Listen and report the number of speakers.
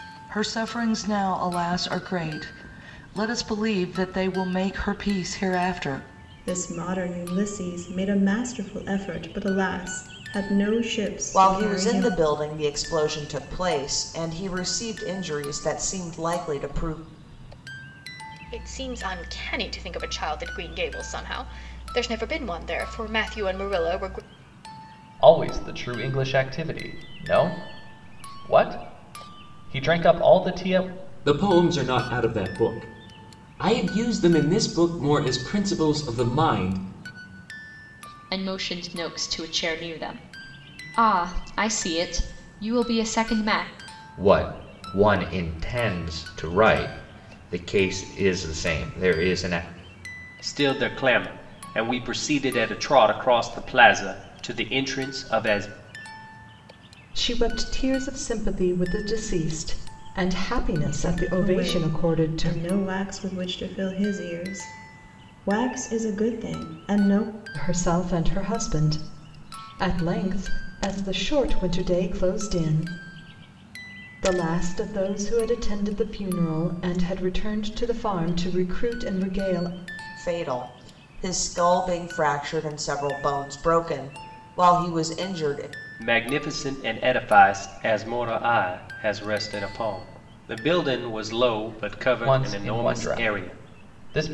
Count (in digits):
10